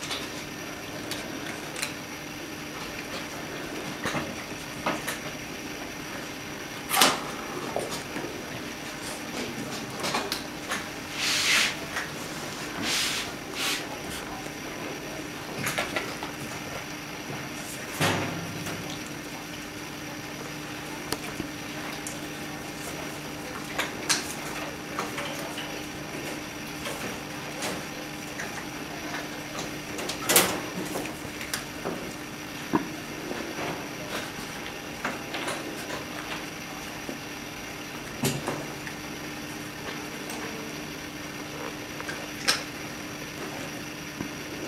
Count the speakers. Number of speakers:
zero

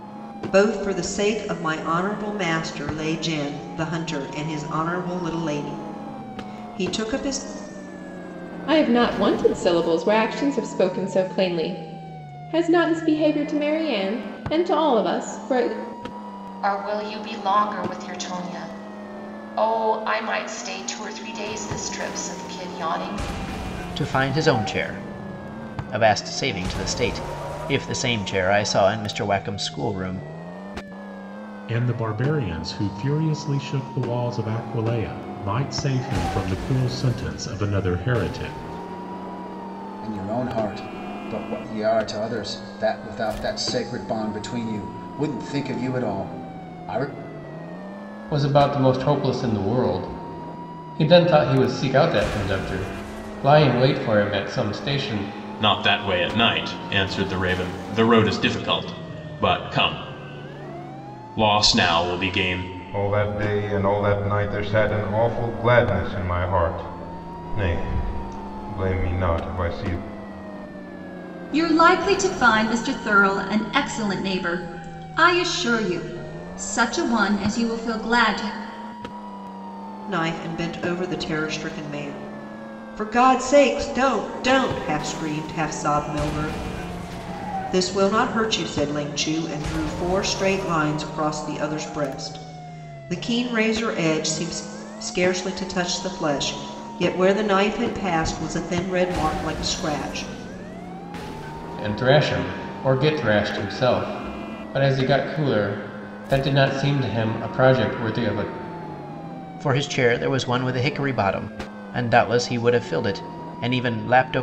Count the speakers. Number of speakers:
ten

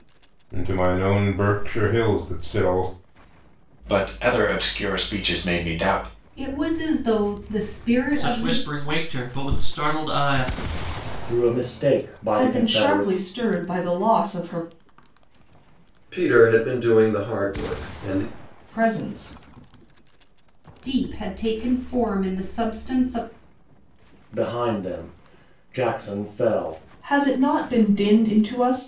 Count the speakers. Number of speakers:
seven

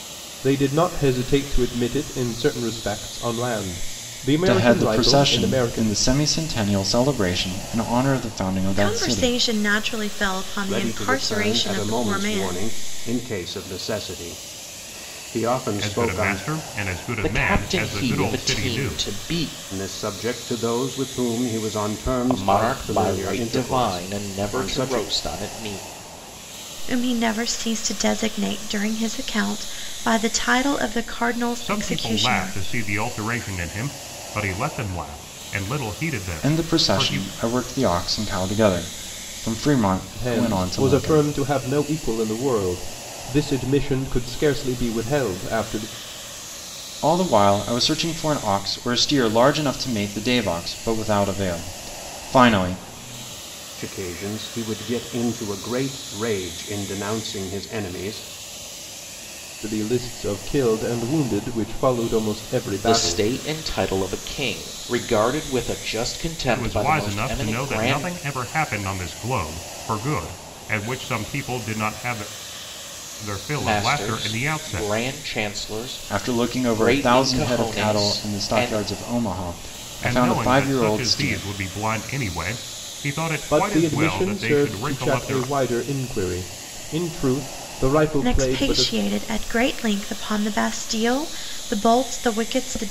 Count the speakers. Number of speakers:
six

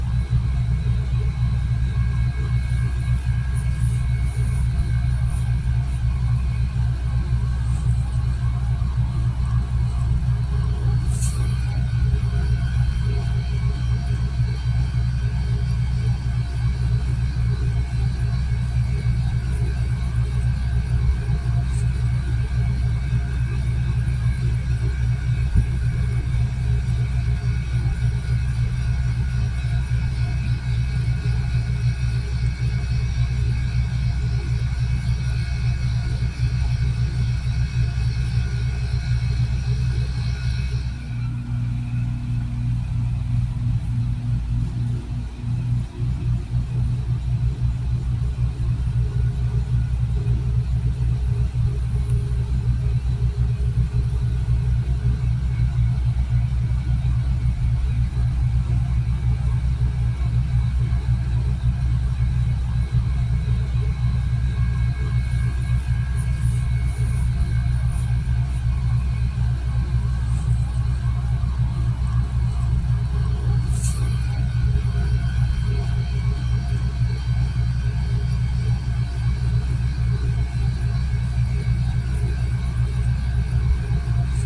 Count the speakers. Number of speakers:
zero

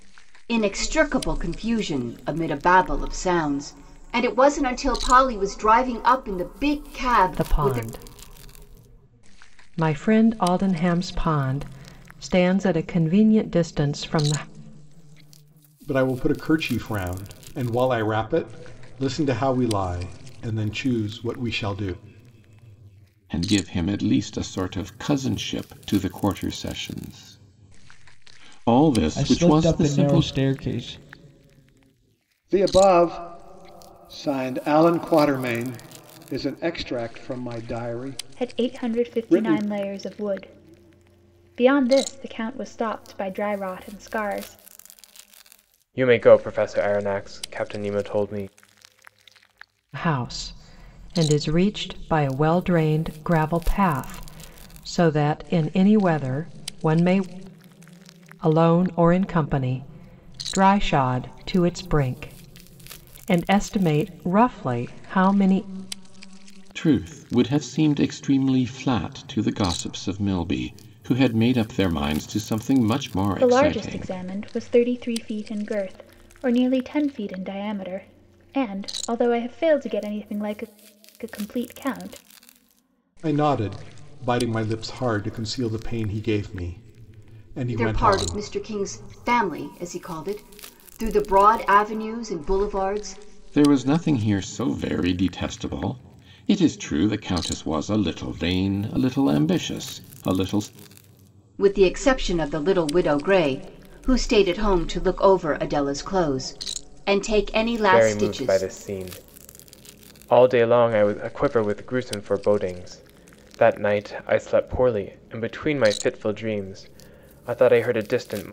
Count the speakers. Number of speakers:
eight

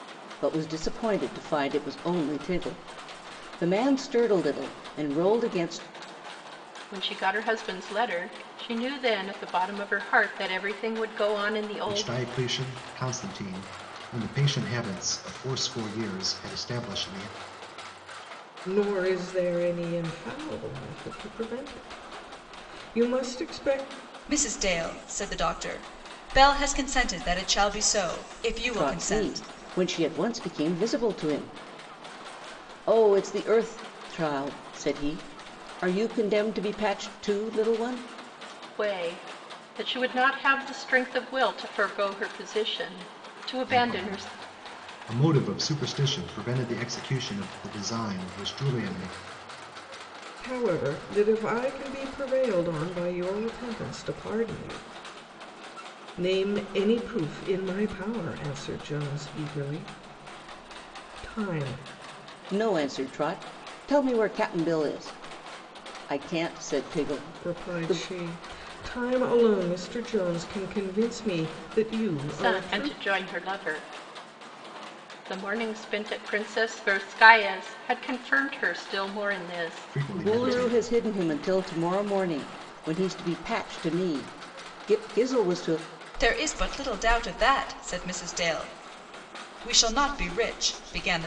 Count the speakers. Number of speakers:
five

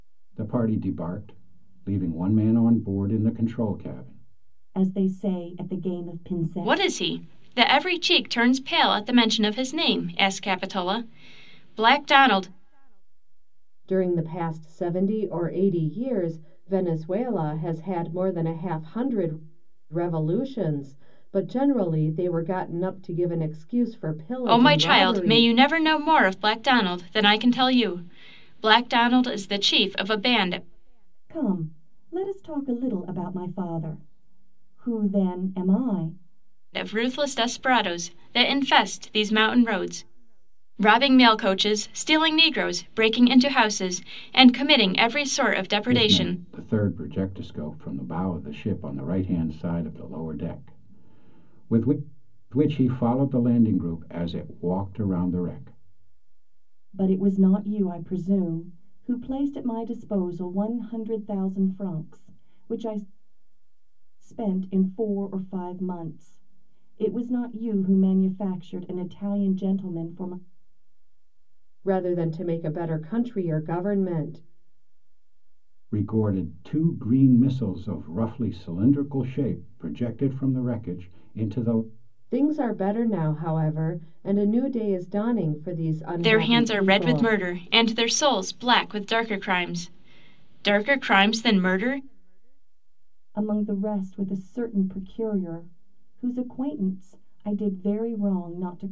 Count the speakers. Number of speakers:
four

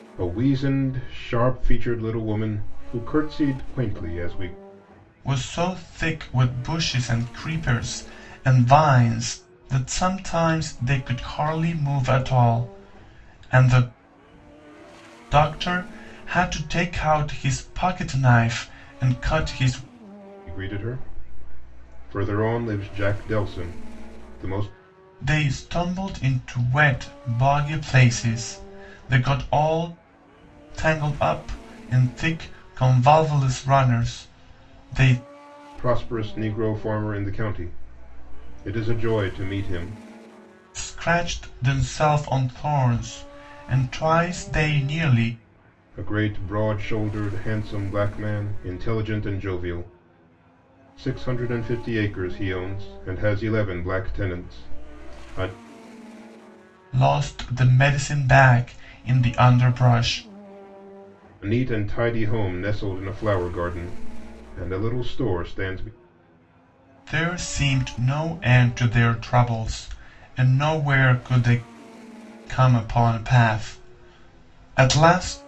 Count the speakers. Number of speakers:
two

